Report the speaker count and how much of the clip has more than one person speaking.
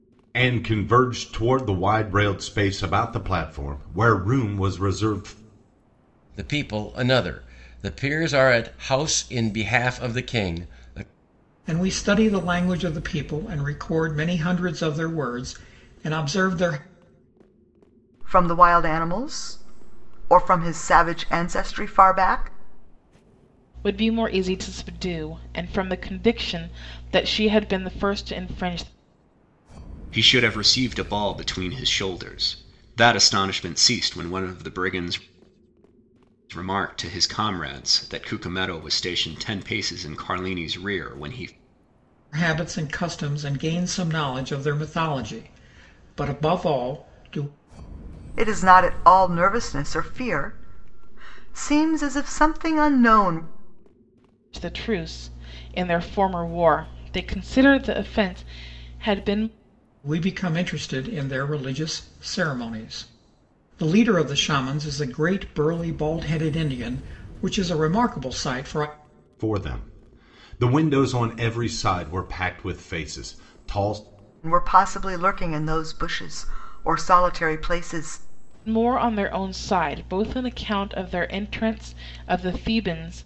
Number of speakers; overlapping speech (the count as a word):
six, no overlap